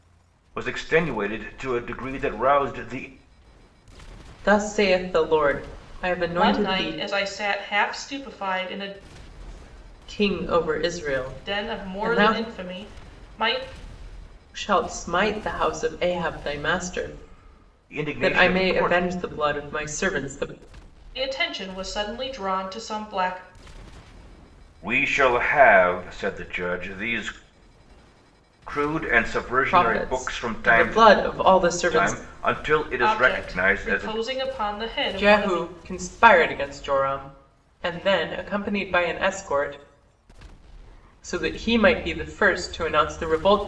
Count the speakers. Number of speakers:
3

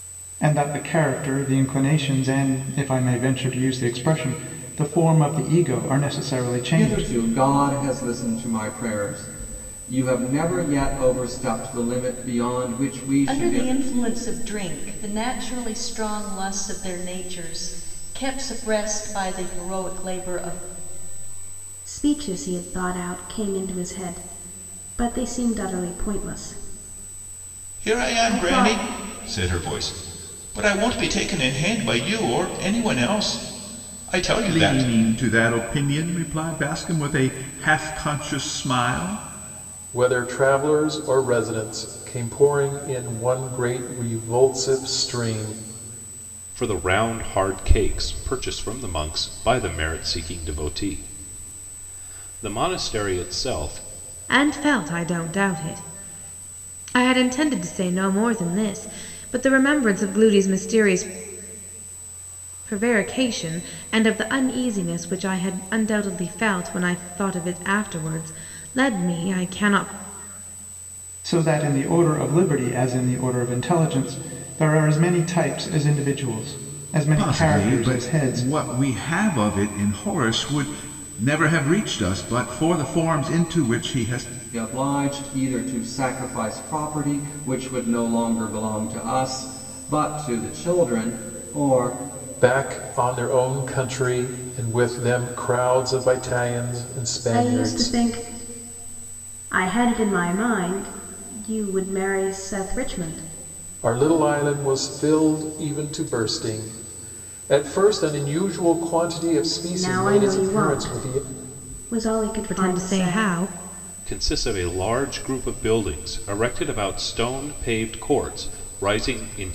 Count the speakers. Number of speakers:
9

